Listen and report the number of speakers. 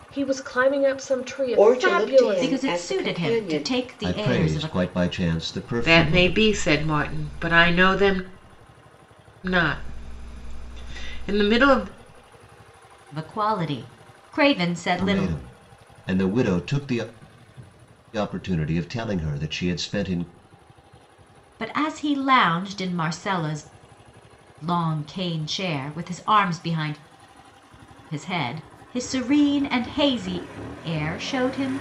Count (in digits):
5